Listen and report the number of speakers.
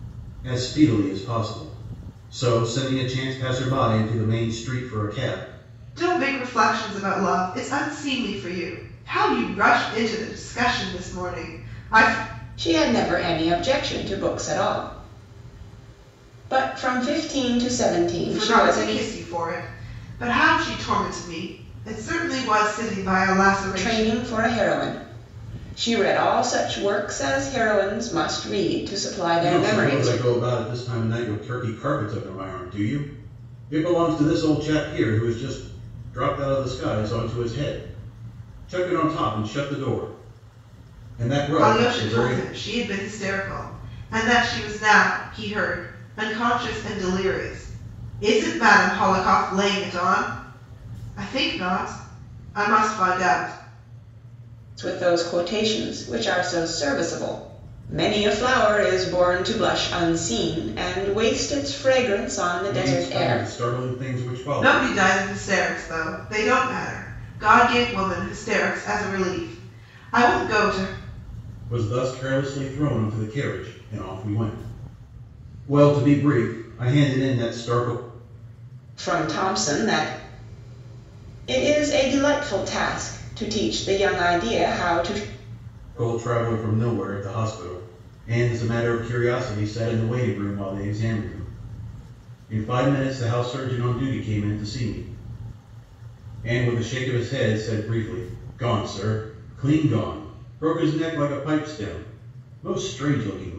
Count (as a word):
three